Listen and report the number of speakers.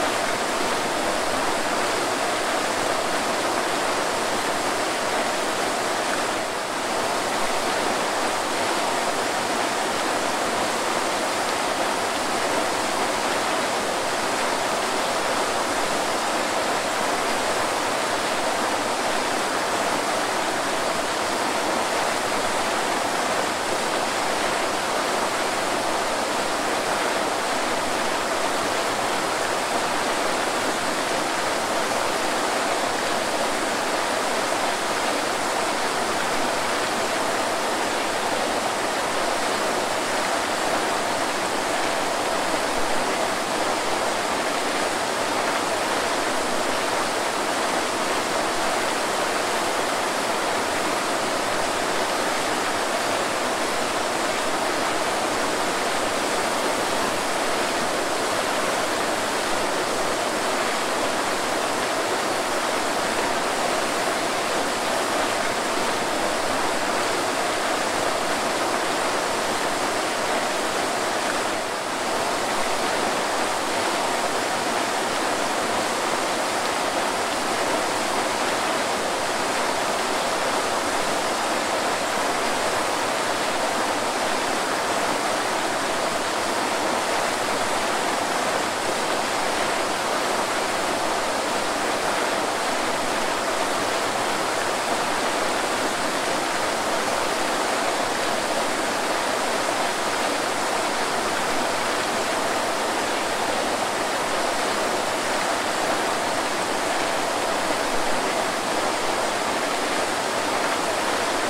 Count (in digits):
0